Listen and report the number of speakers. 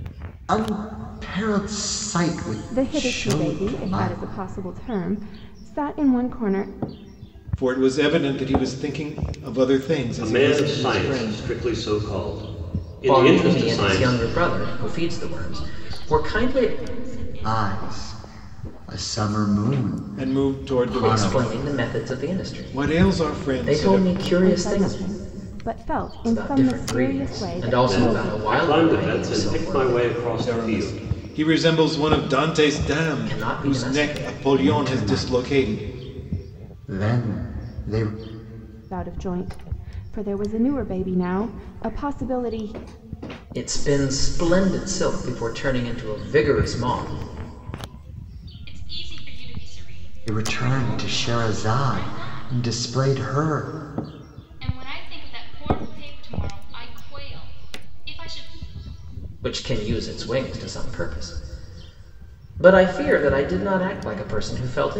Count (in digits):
6